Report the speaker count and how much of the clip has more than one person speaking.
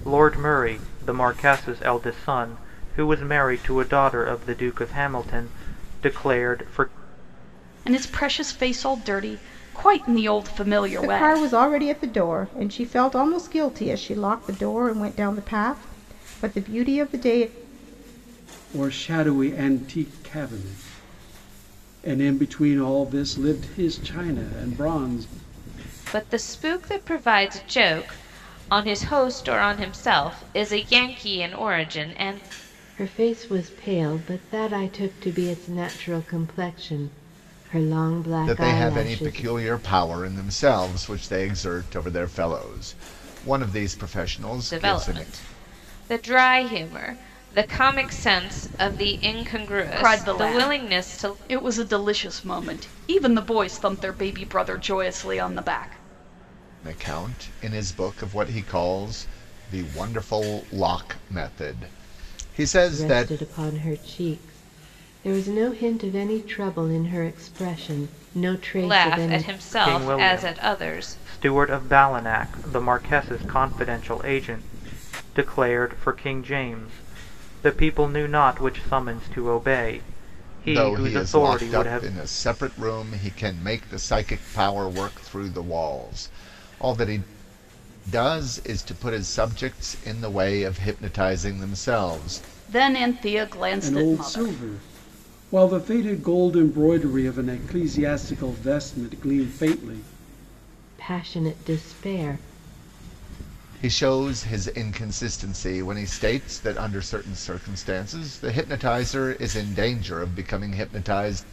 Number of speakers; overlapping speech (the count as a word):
seven, about 8%